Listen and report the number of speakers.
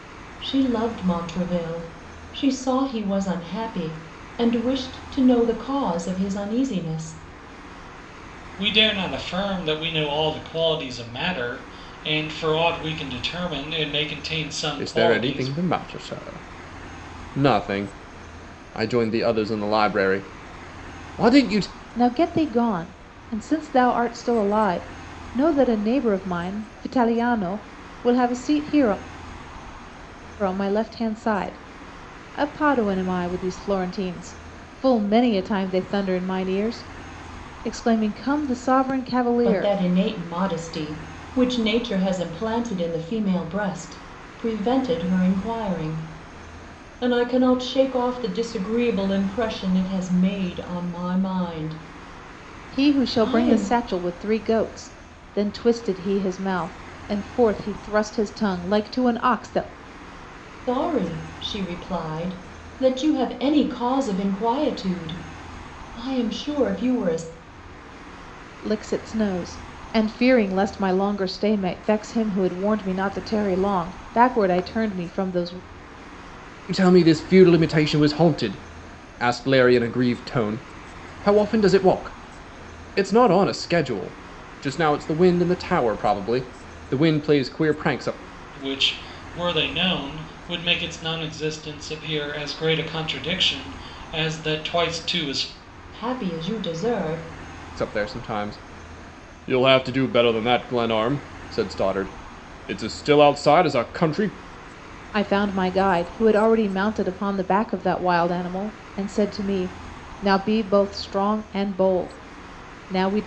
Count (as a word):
four